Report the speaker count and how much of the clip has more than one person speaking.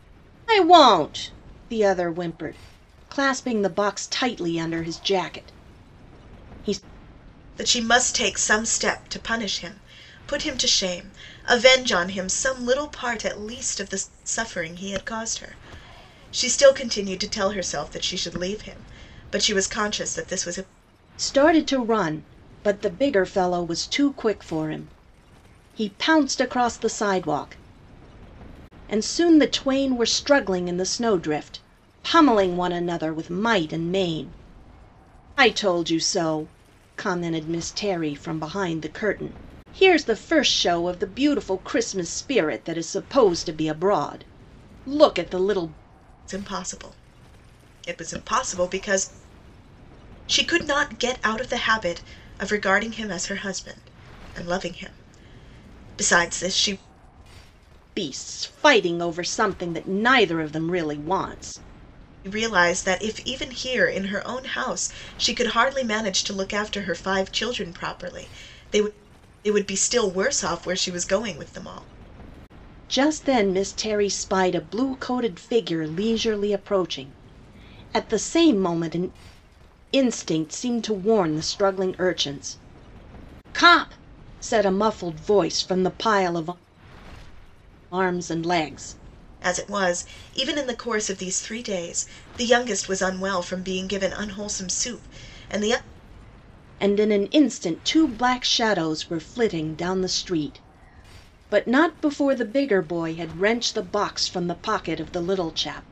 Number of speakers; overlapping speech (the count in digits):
2, no overlap